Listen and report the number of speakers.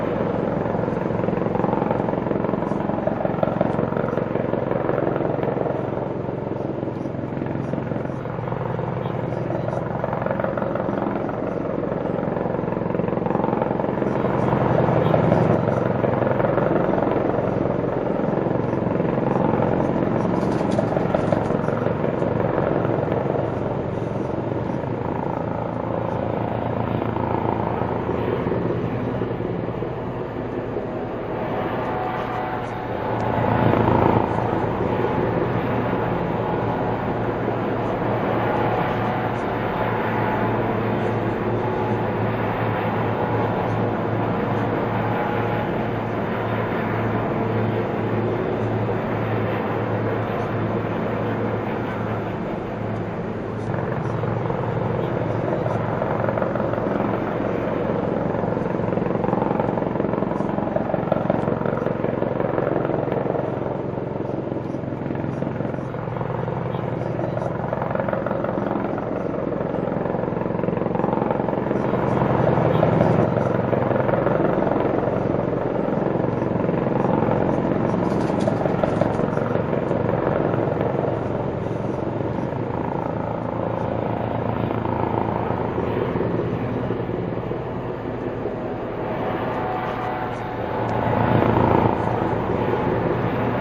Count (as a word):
zero